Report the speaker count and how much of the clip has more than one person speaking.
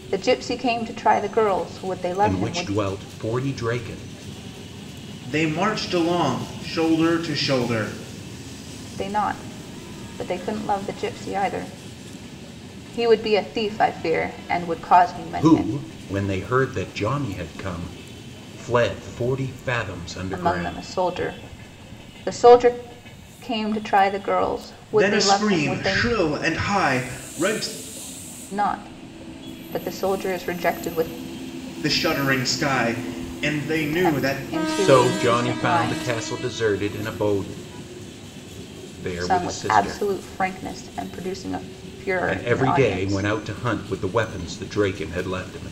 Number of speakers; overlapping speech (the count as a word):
three, about 15%